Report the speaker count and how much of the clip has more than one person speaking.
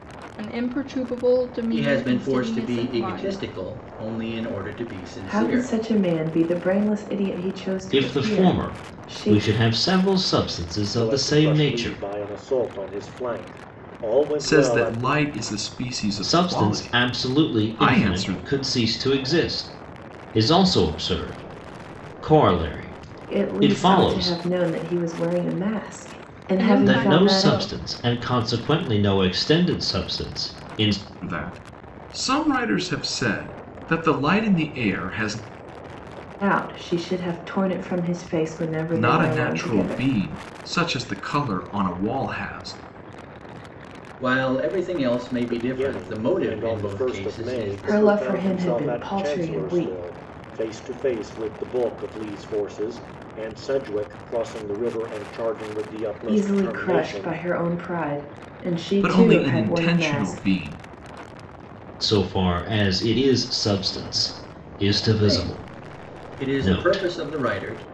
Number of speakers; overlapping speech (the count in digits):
6, about 30%